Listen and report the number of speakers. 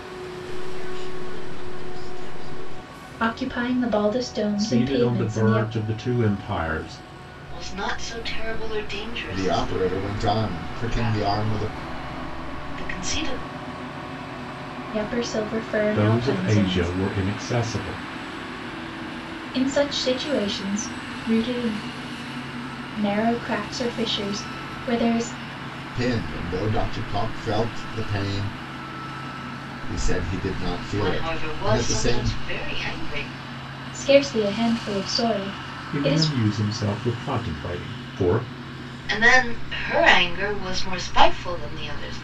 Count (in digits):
5